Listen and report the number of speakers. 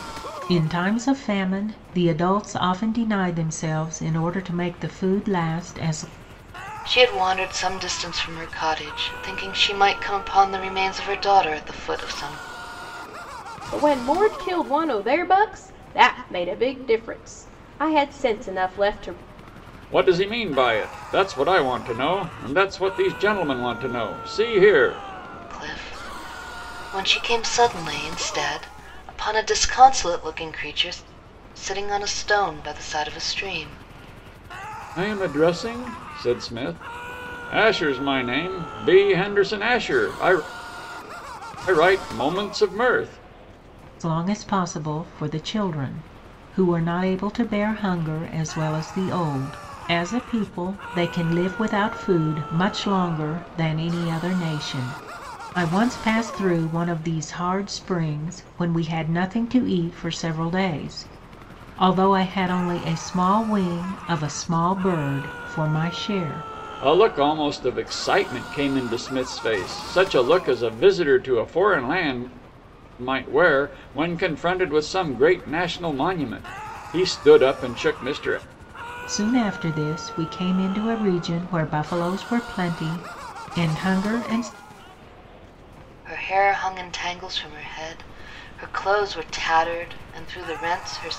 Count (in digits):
4